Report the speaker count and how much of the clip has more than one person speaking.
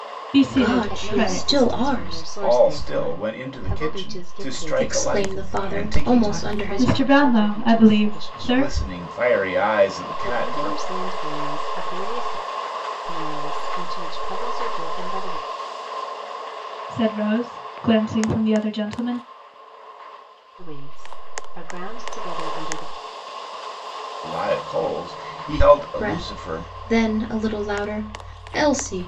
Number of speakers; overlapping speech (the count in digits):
4, about 31%